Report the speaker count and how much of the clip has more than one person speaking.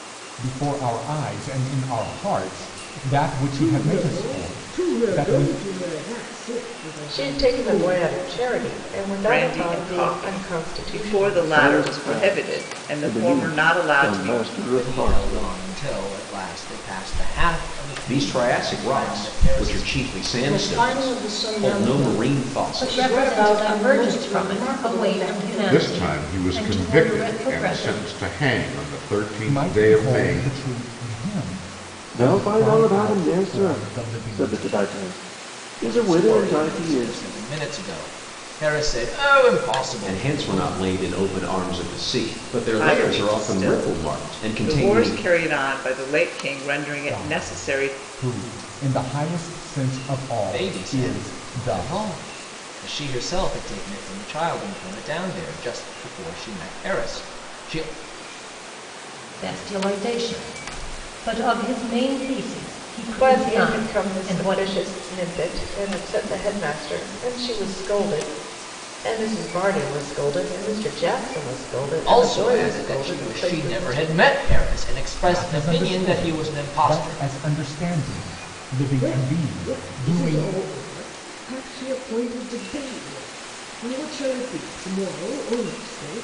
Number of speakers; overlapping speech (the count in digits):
10, about 43%